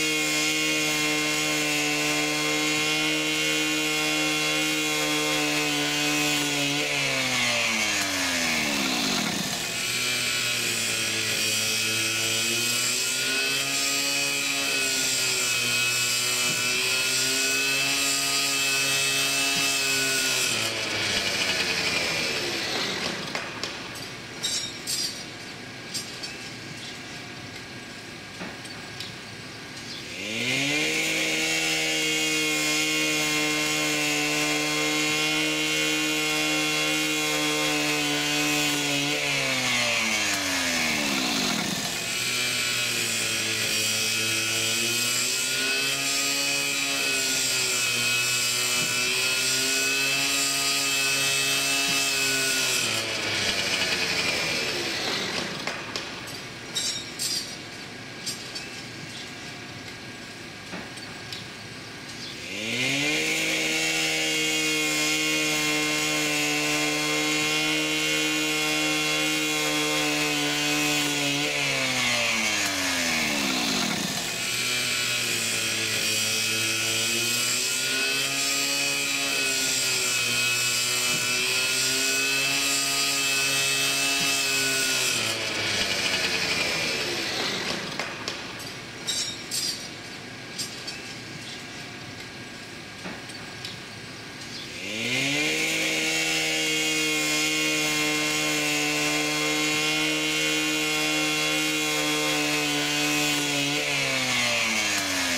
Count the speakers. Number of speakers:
zero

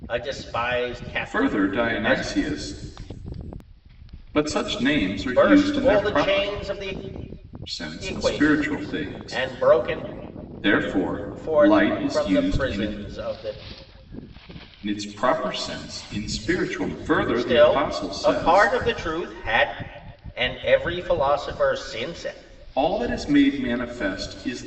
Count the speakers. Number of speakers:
two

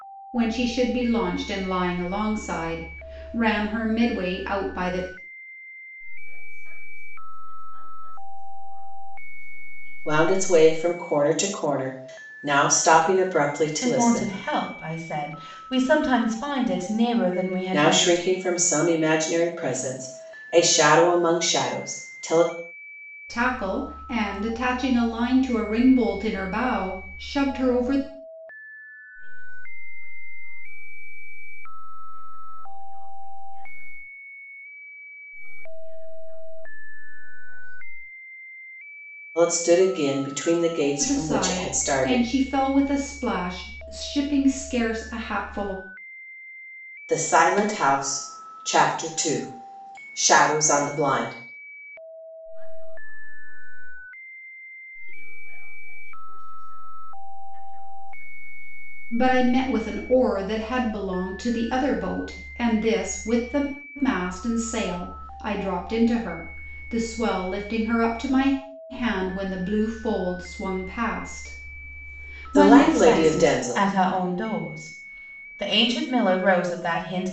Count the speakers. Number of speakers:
four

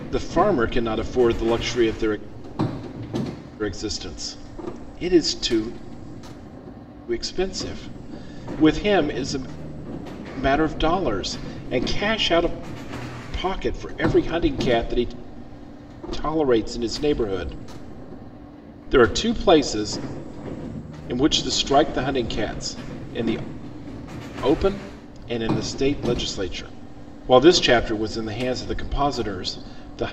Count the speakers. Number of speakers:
one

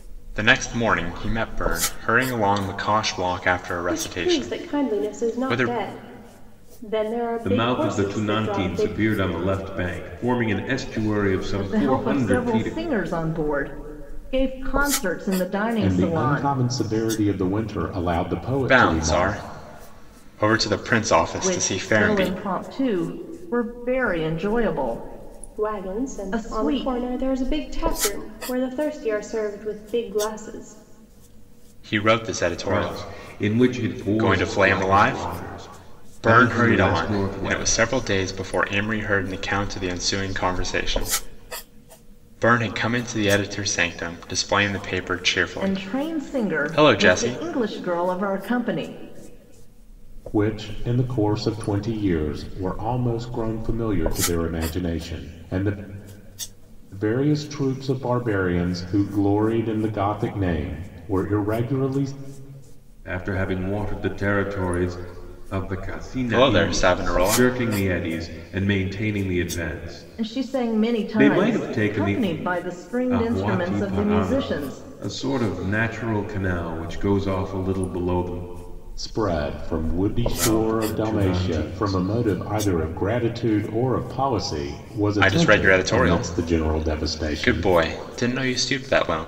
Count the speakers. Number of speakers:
five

